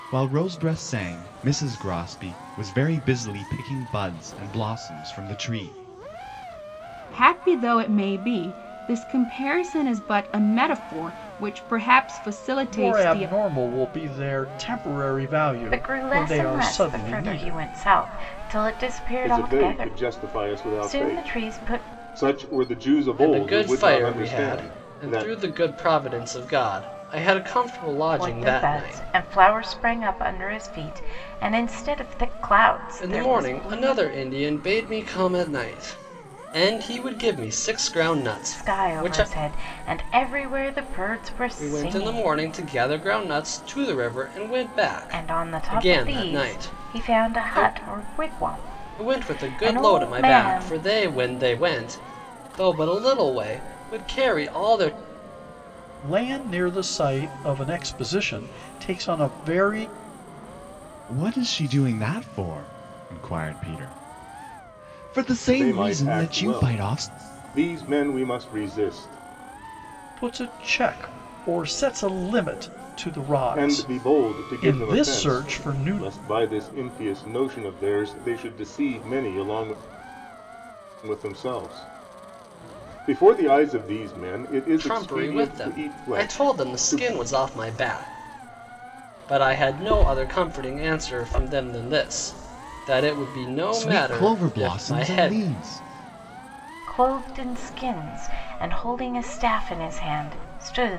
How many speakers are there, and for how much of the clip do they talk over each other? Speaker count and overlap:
6, about 24%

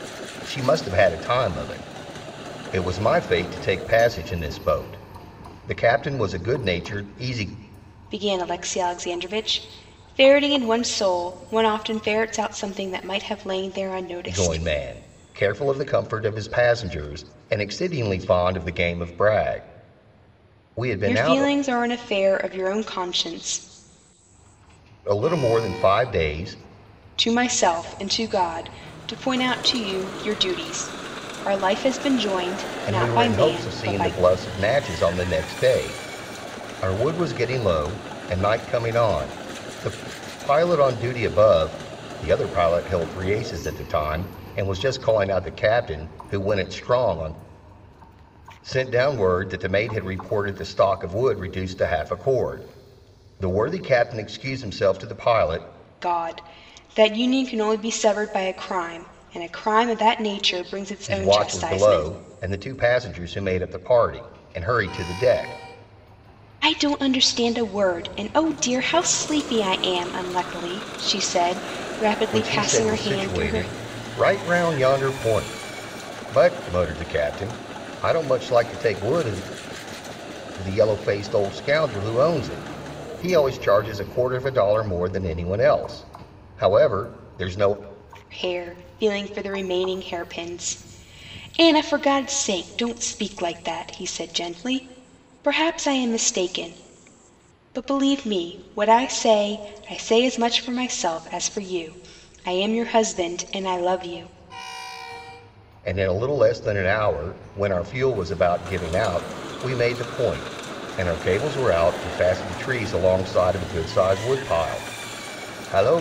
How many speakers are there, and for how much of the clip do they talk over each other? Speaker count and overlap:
2, about 4%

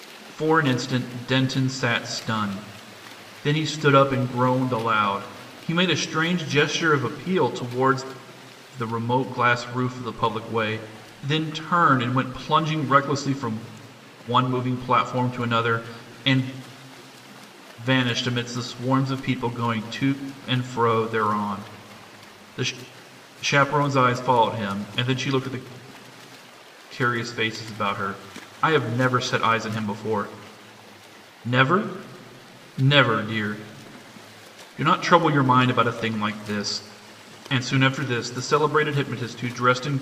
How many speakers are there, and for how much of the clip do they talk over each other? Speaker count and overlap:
1, no overlap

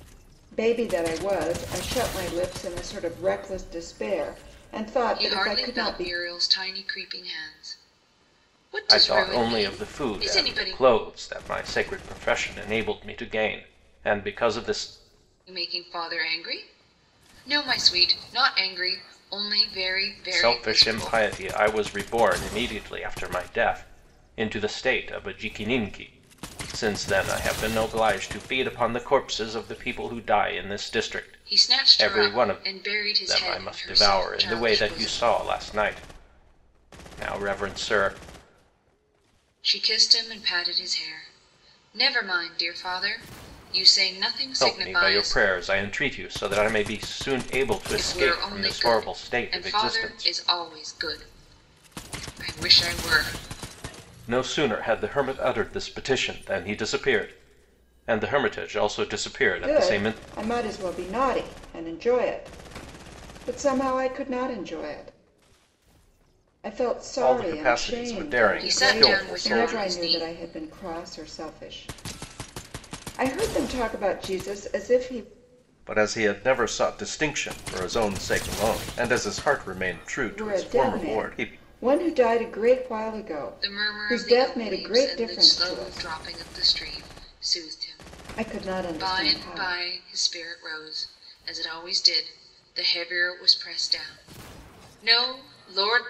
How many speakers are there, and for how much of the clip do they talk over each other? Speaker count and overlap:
3, about 20%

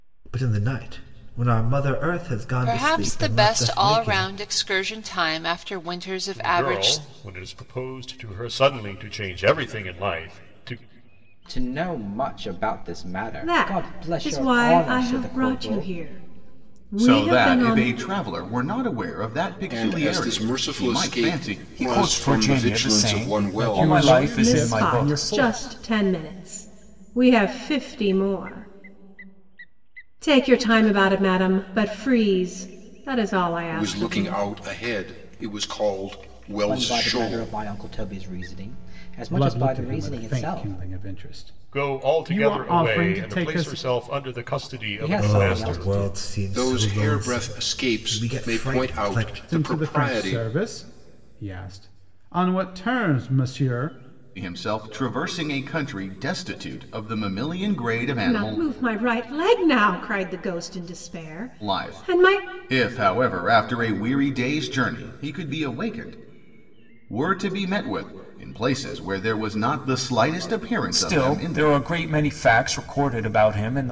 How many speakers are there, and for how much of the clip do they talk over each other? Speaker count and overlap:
9, about 33%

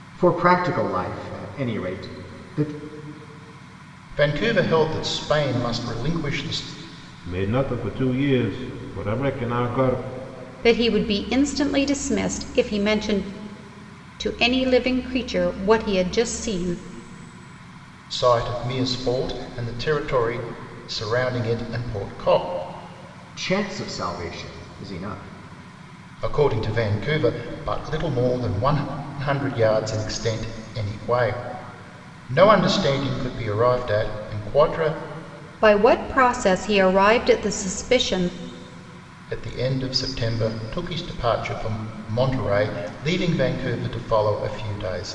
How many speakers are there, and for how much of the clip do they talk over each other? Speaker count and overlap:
4, no overlap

